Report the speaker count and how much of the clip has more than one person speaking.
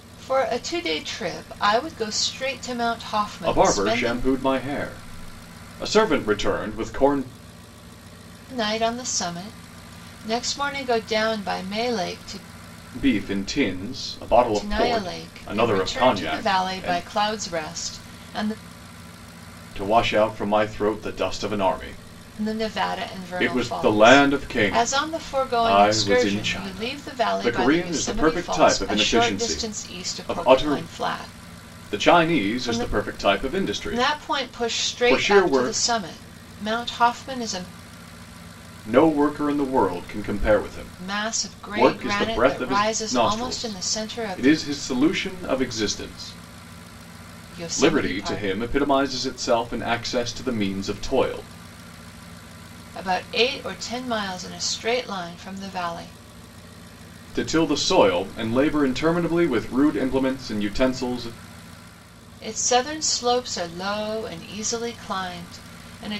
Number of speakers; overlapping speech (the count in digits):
2, about 28%